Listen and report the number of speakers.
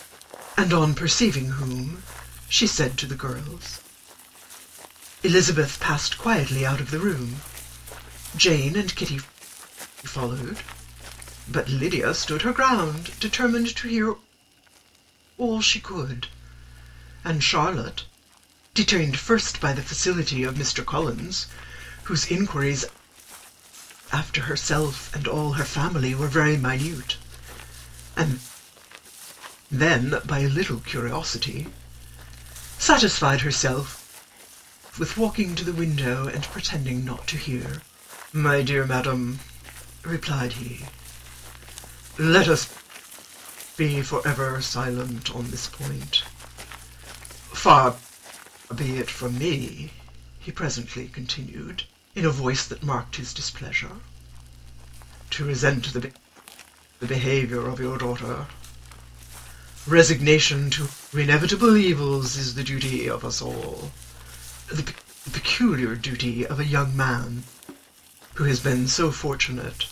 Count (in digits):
1